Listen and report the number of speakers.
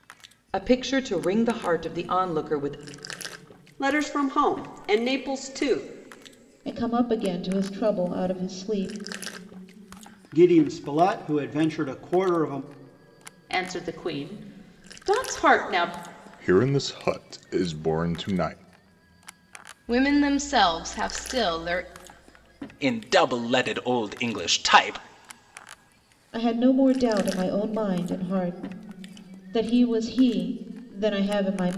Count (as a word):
eight